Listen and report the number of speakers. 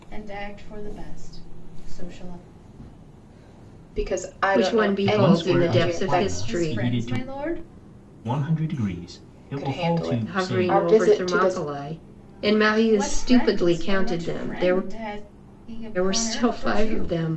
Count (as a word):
four